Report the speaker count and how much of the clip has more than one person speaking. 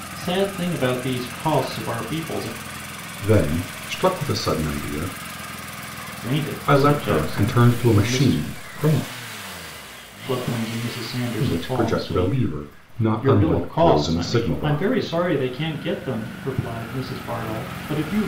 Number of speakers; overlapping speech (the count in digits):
2, about 25%